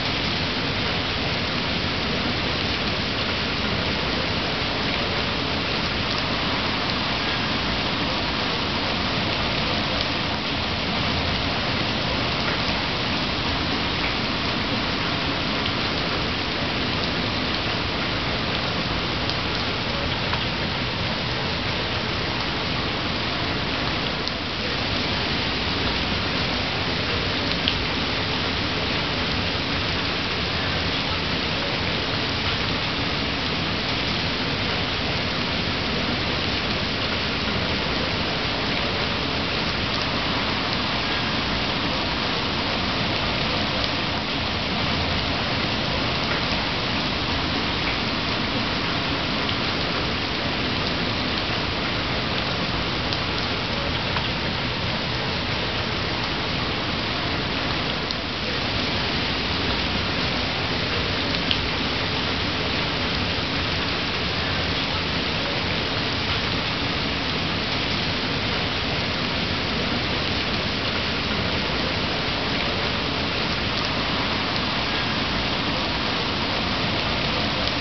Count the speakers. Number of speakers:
0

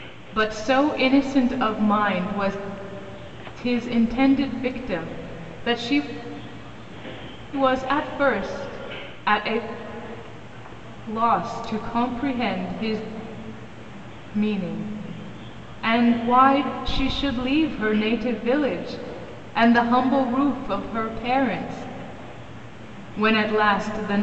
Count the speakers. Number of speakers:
1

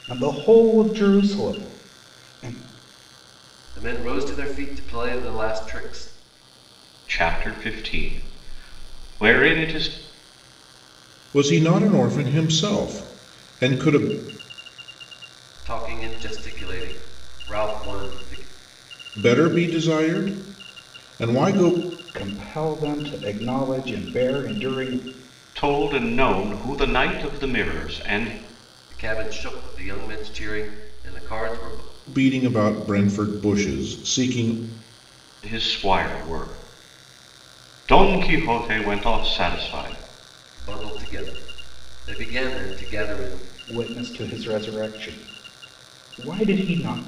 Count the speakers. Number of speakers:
4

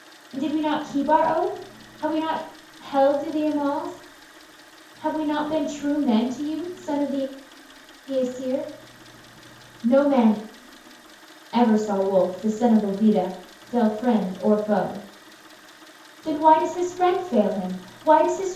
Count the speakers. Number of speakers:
1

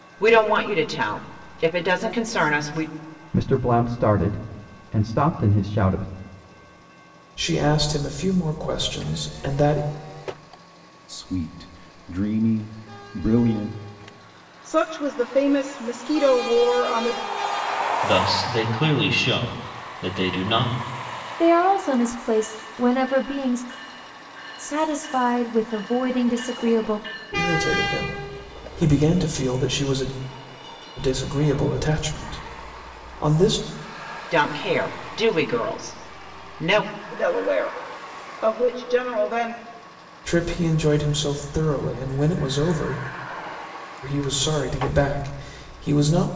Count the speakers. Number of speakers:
7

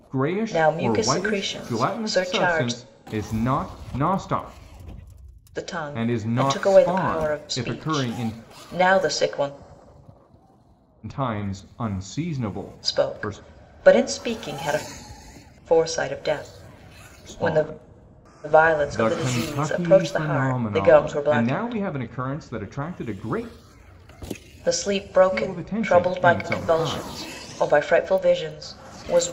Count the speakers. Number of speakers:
2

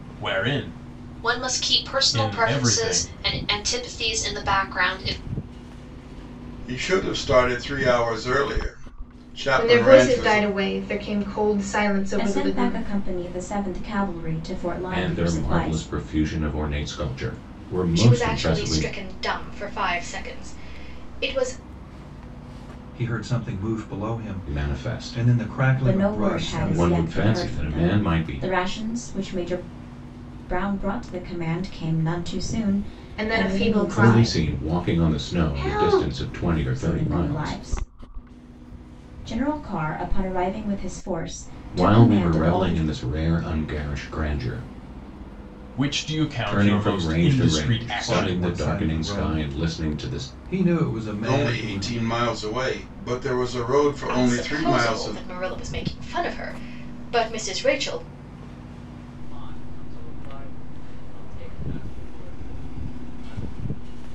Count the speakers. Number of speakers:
9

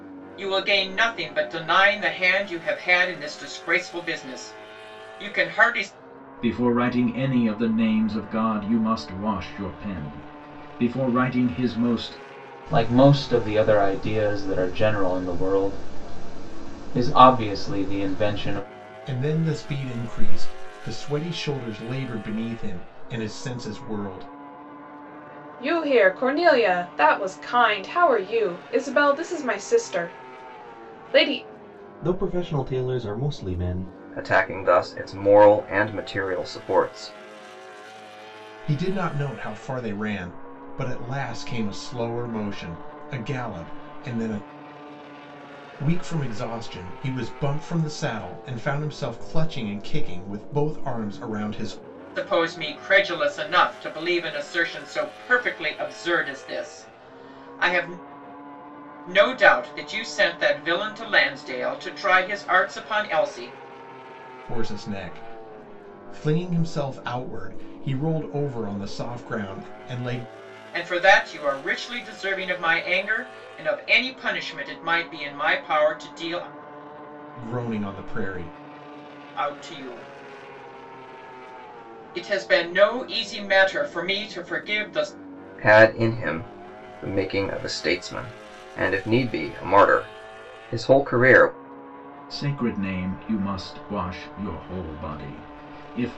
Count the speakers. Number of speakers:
7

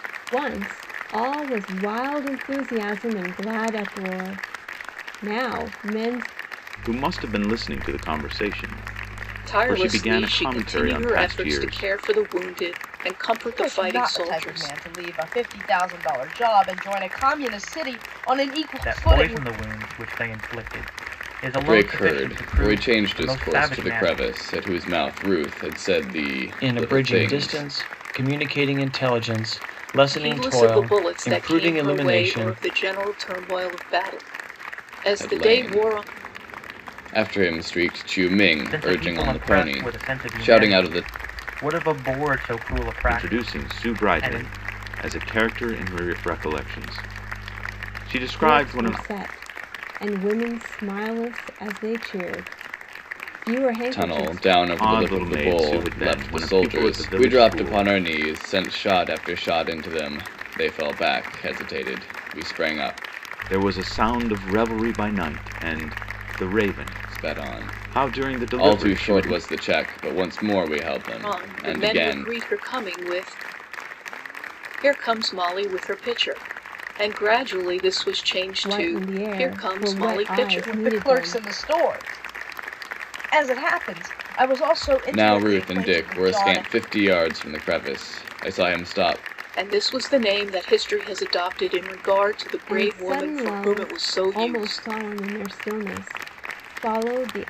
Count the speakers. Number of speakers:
7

